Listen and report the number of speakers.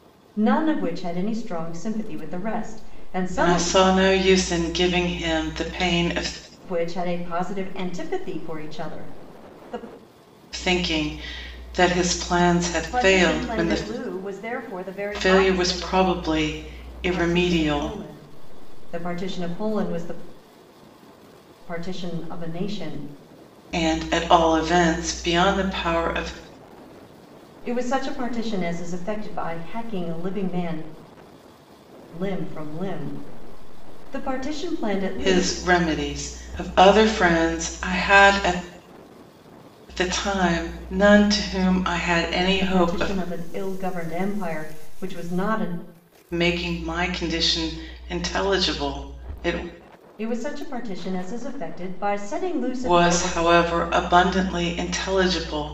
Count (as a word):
two